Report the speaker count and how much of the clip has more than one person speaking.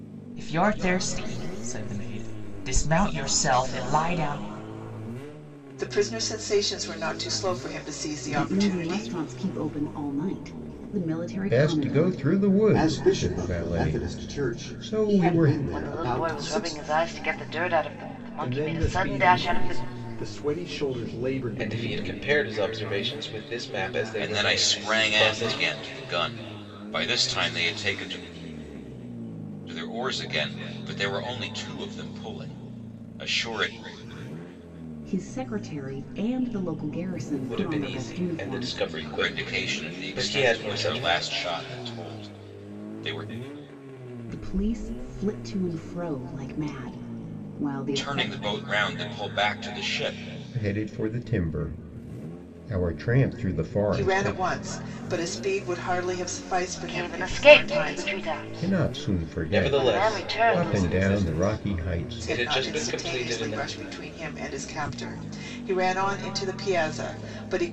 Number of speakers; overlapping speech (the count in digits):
9, about 30%